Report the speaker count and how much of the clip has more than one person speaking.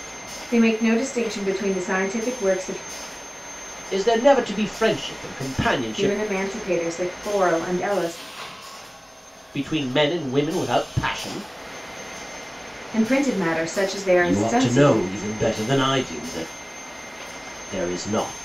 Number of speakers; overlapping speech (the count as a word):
two, about 7%